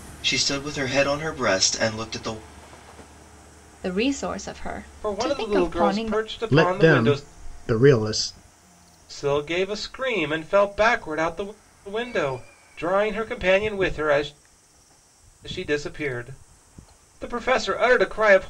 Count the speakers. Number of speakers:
four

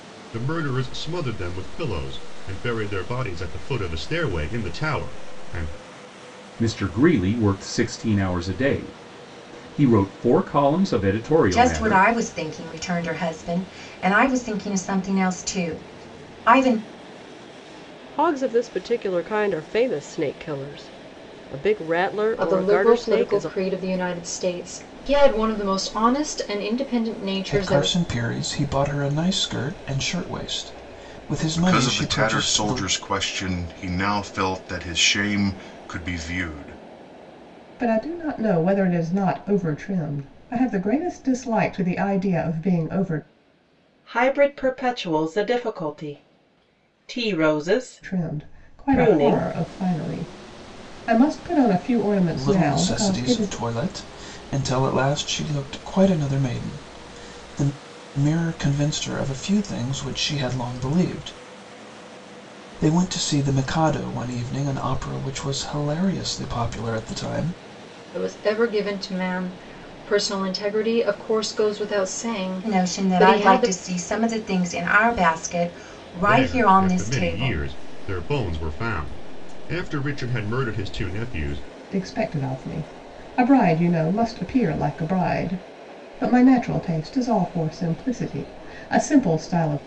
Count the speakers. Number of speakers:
nine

